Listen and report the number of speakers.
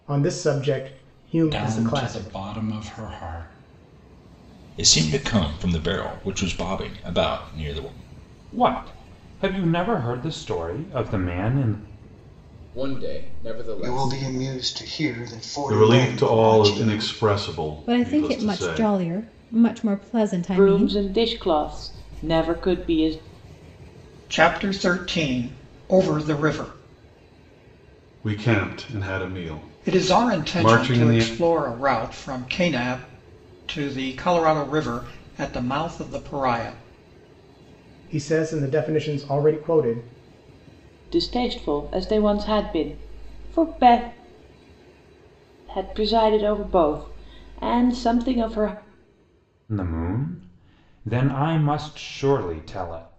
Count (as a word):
ten